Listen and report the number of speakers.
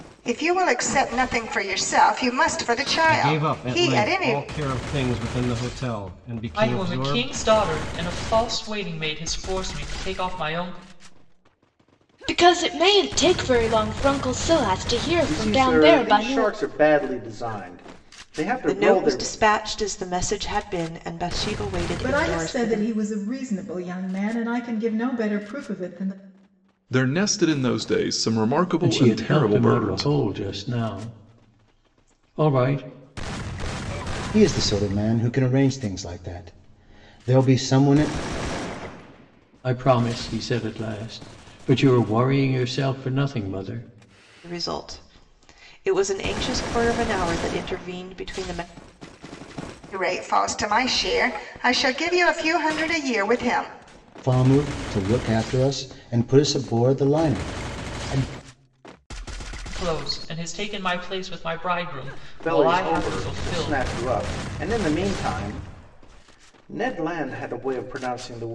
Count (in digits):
10